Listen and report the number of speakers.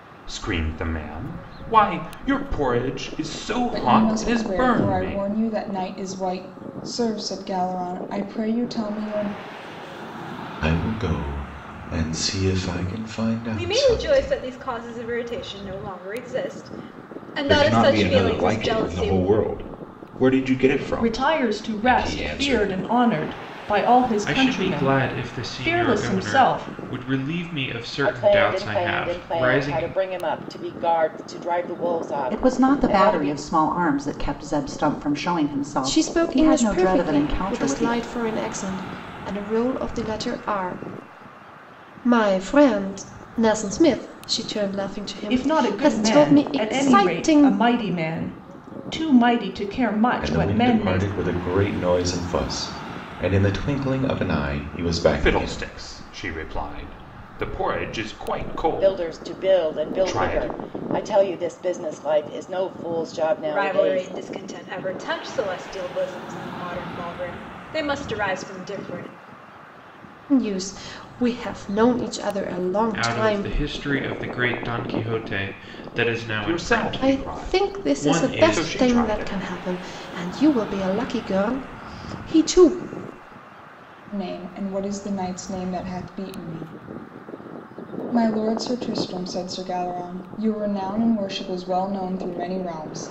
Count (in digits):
10